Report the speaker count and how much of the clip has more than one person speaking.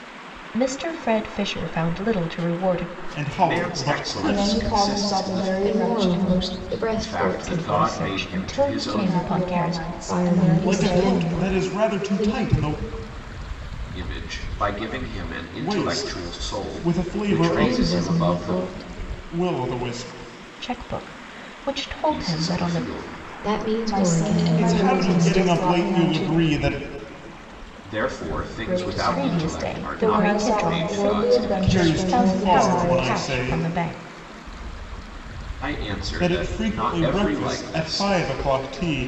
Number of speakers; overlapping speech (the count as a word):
five, about 56%